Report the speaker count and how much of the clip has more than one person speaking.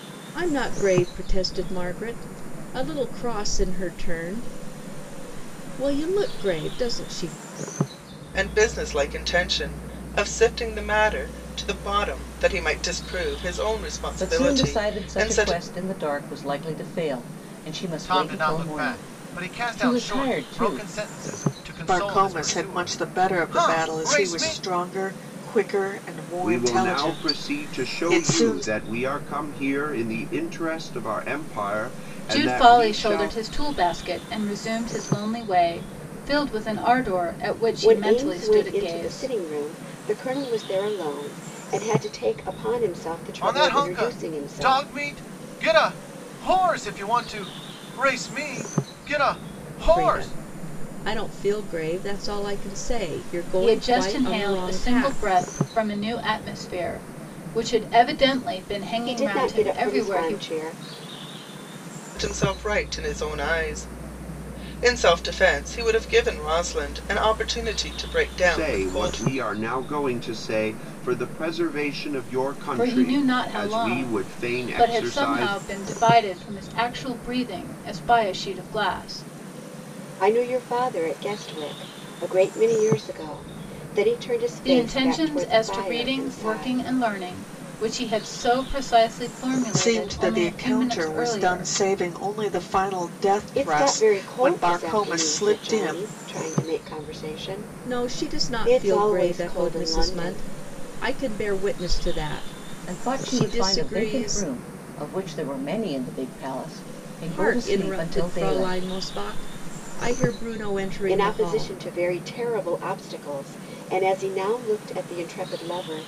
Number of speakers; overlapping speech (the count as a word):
eight, about 30%